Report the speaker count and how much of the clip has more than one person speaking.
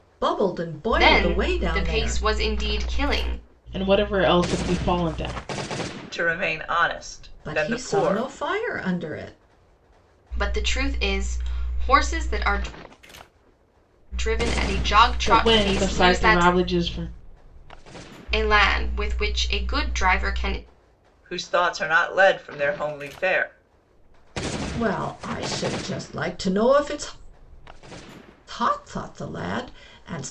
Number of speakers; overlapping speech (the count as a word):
four, about 12%